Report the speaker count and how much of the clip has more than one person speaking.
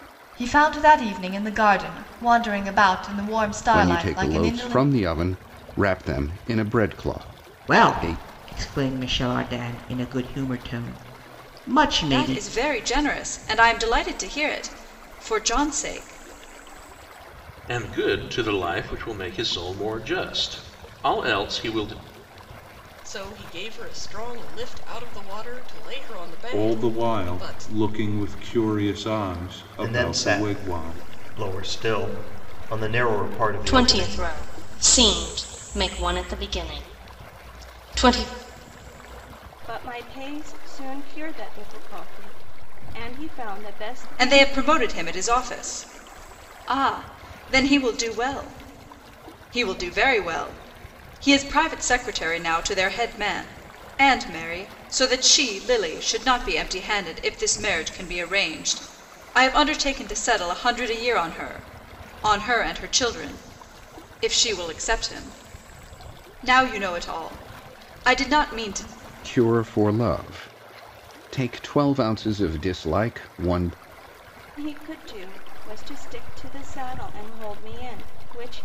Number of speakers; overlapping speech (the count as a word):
ten, about 7%